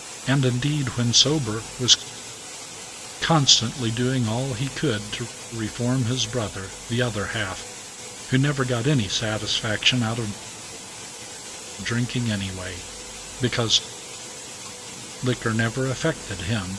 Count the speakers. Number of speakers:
one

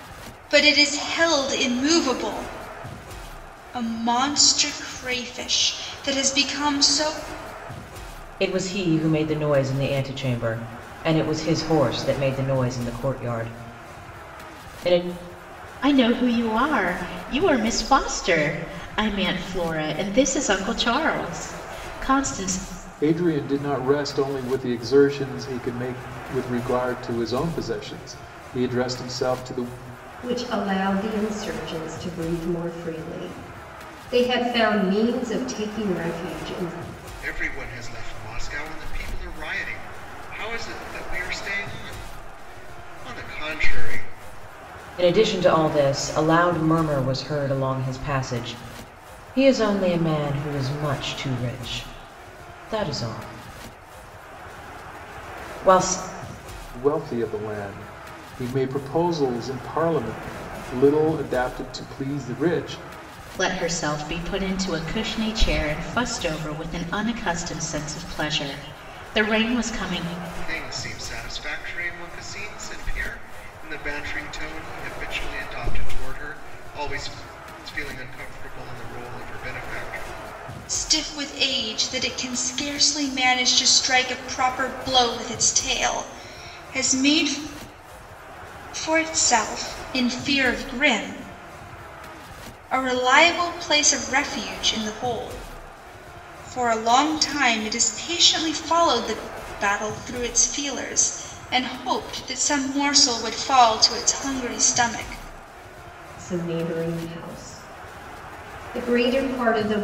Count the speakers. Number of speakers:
six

